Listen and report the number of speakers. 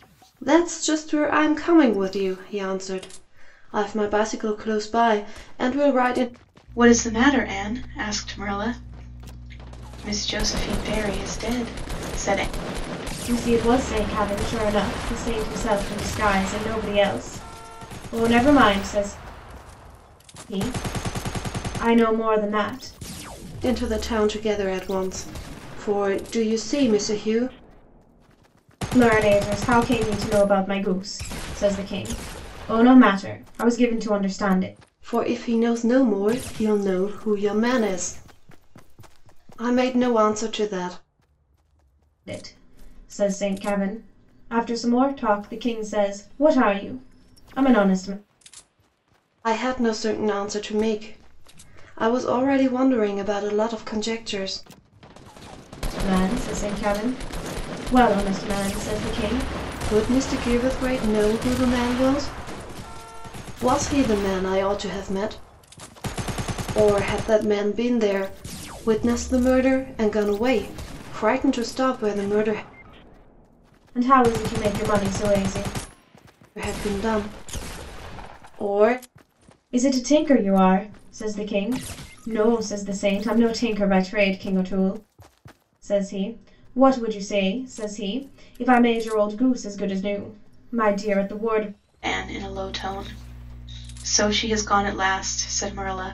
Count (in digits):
3